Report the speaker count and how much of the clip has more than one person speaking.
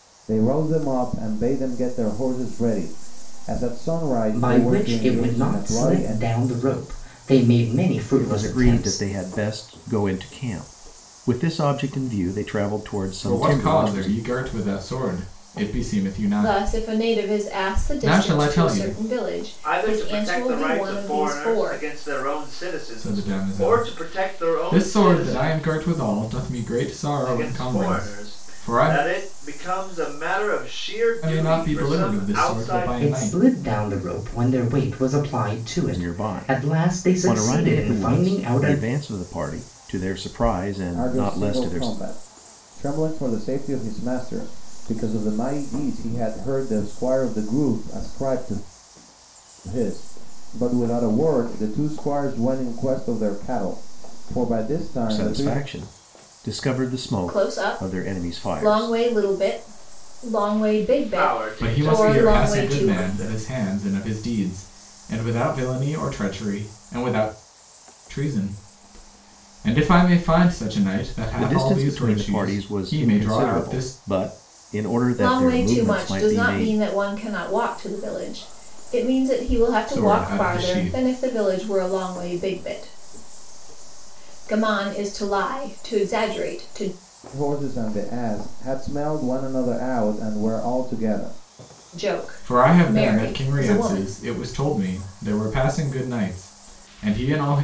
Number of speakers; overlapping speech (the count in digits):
6, about 32%